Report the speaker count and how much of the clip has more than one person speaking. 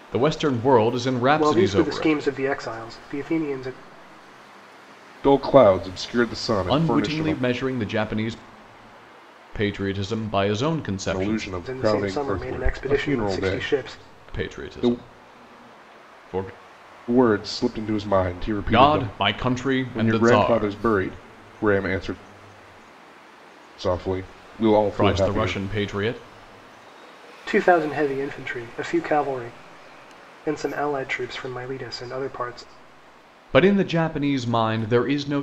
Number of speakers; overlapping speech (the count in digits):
3, about 20%